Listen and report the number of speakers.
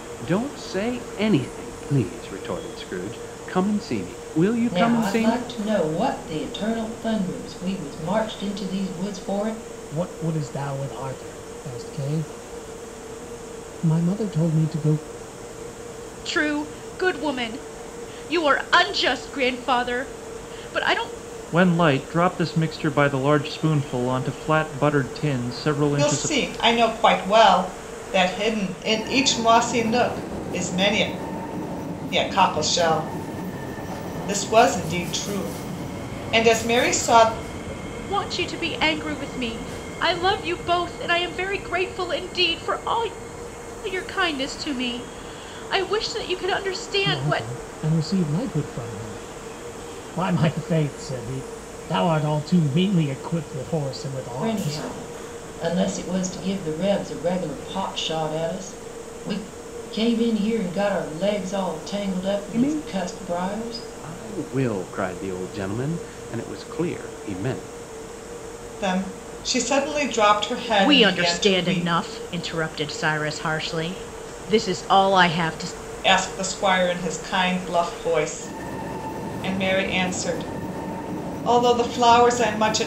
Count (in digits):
6